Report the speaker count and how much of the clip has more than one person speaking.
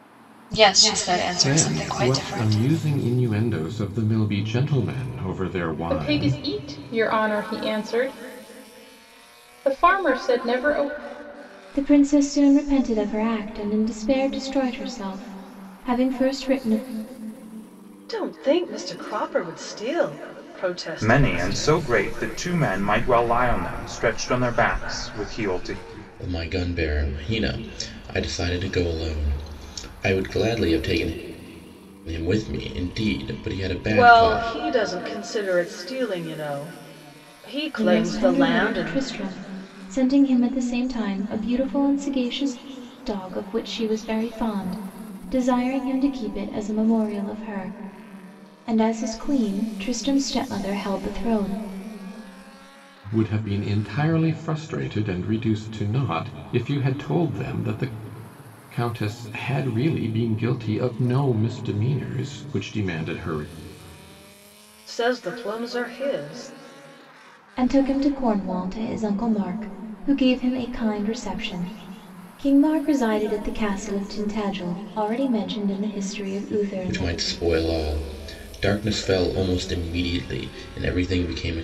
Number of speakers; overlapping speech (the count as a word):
seven, about 6%